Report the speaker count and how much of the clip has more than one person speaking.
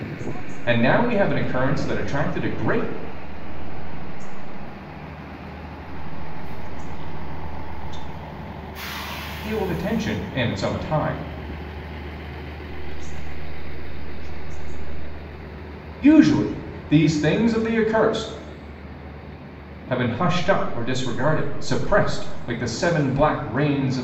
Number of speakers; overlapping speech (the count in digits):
2, about 19%